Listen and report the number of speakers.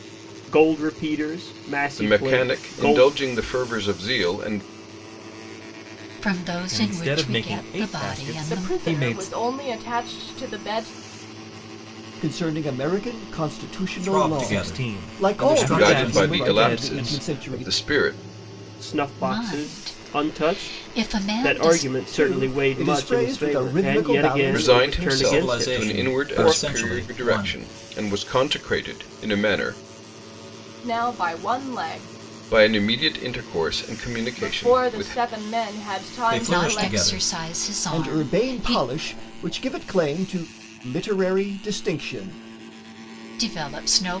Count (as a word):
seven